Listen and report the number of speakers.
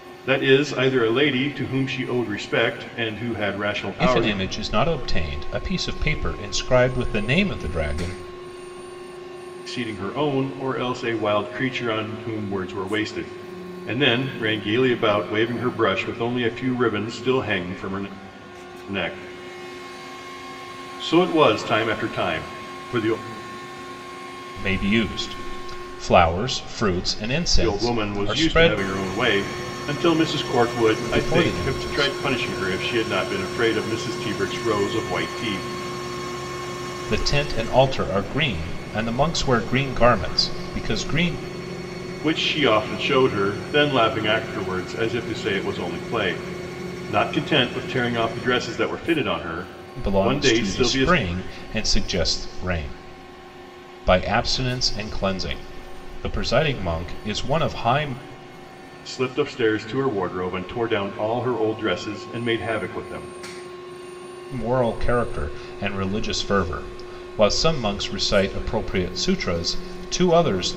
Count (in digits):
2